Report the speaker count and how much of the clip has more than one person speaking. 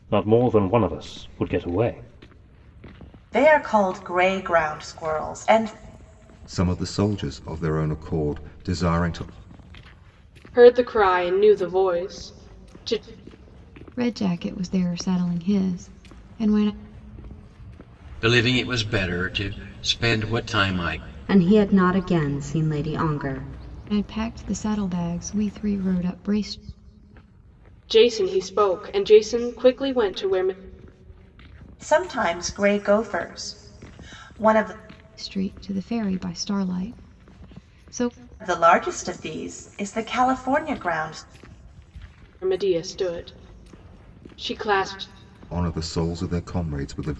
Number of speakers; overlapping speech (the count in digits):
7, no overlap